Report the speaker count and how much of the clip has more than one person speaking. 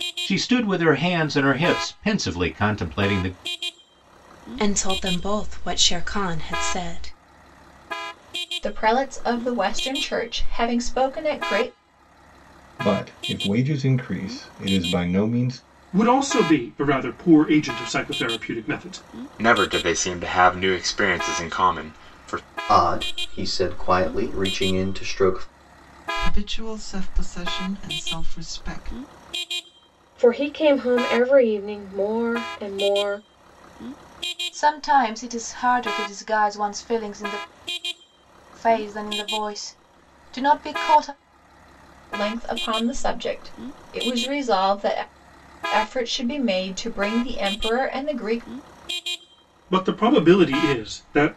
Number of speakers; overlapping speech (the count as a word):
ten, no overlap